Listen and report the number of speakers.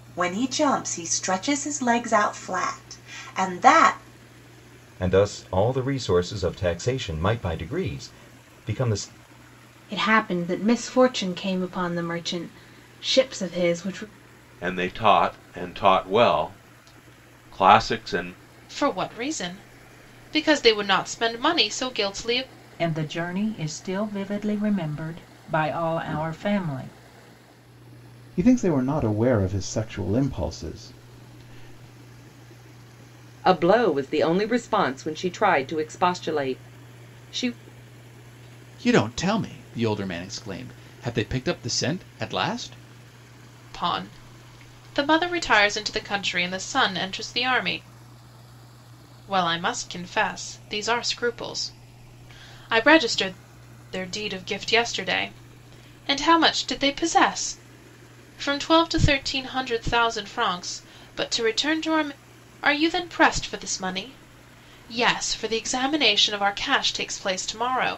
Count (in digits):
9